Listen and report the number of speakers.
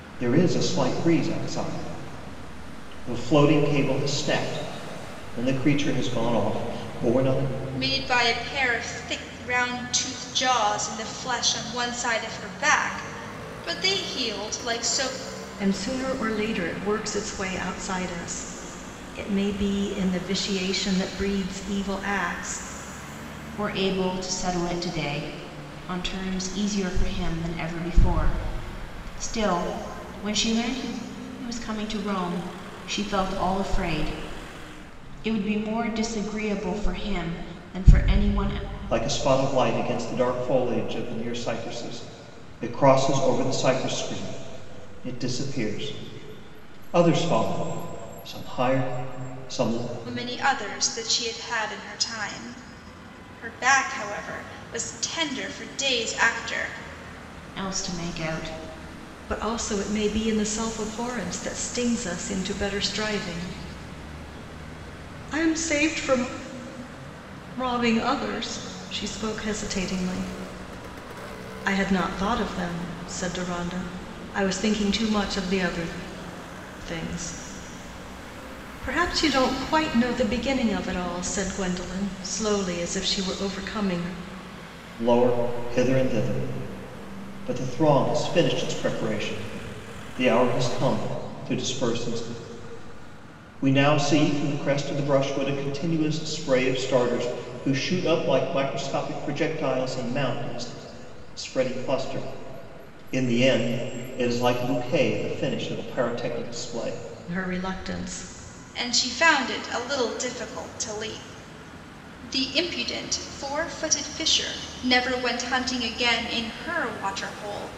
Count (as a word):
four